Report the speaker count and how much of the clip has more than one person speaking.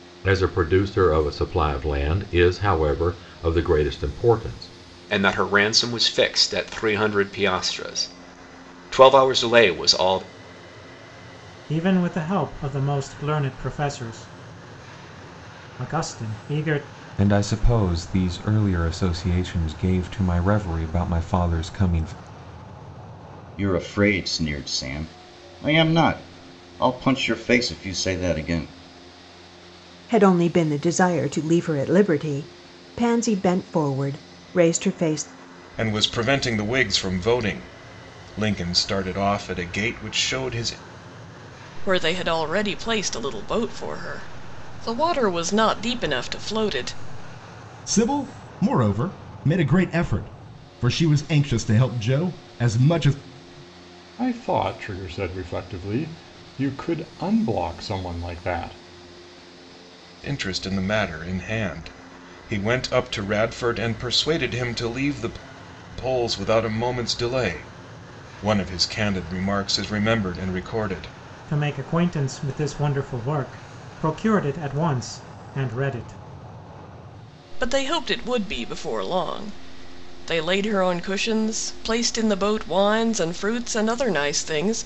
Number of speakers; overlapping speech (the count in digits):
10, no overlap